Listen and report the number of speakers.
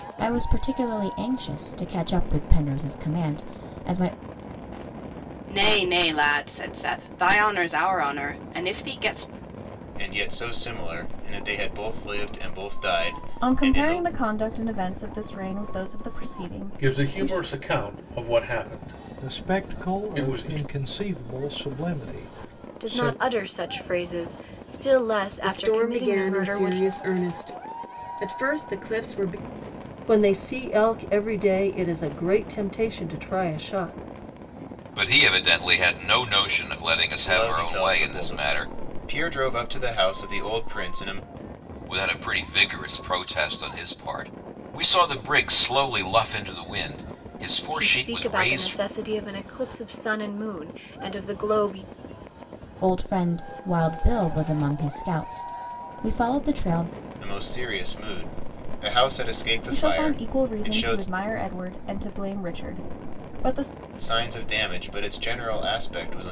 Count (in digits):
10